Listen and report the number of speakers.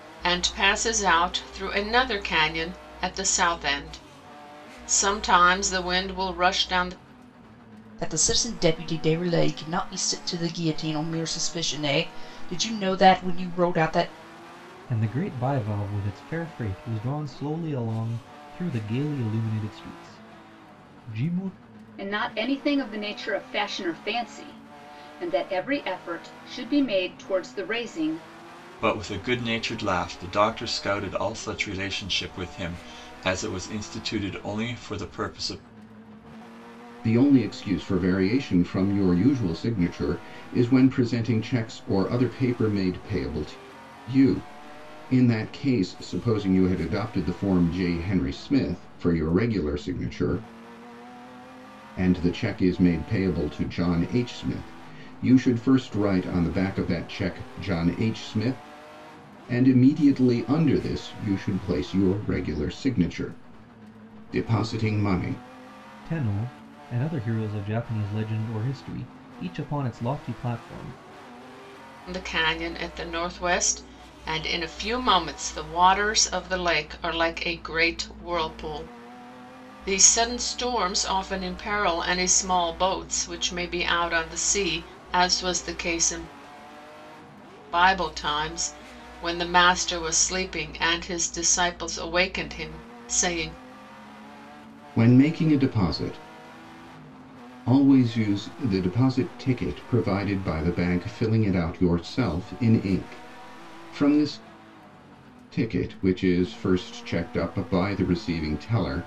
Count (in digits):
6